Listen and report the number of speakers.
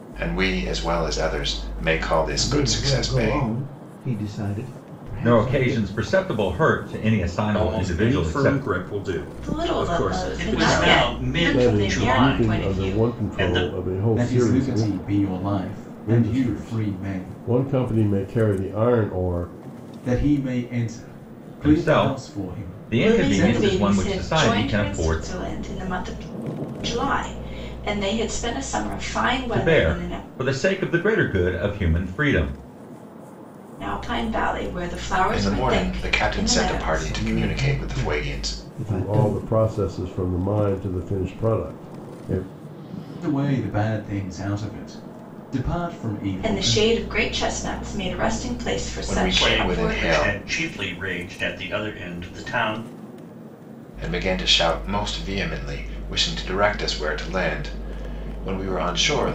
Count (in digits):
8